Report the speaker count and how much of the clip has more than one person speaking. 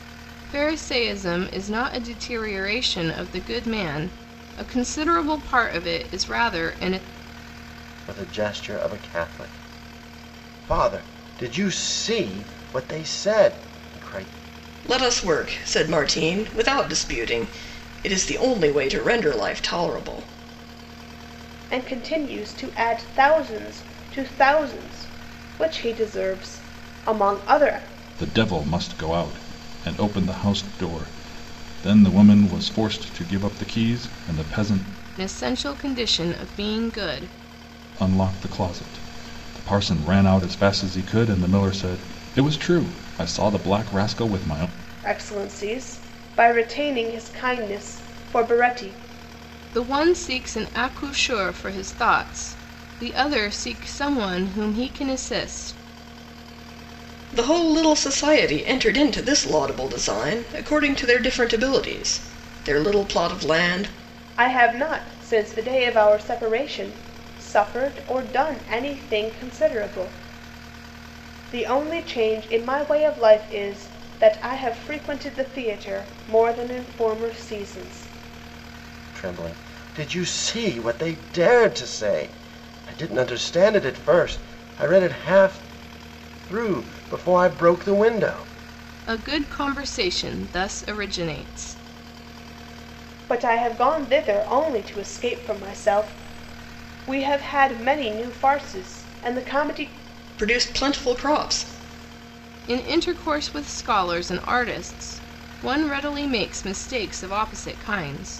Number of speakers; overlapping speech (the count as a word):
five, no overlap